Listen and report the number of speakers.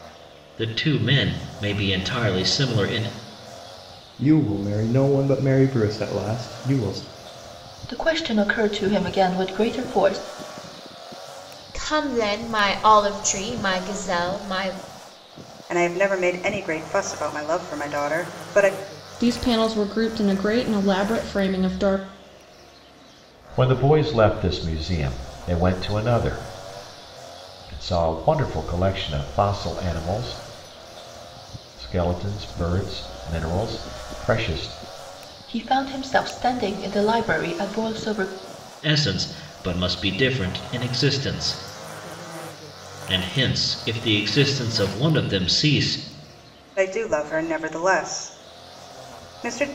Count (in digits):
7